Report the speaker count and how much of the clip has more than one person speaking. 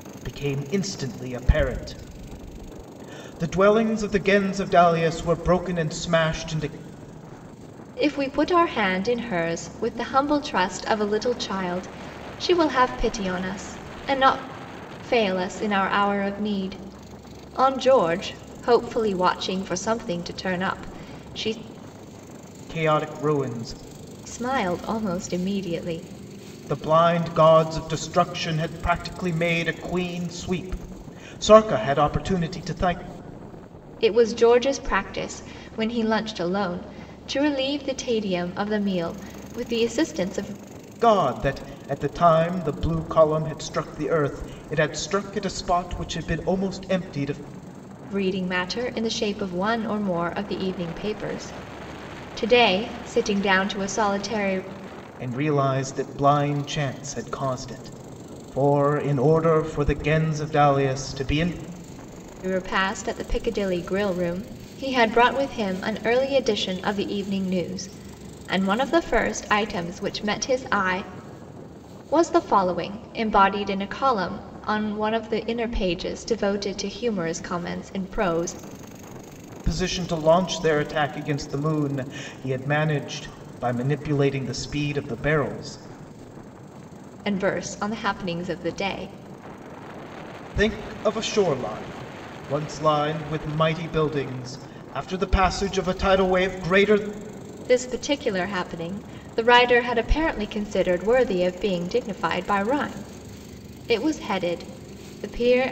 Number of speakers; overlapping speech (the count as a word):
two, no overlap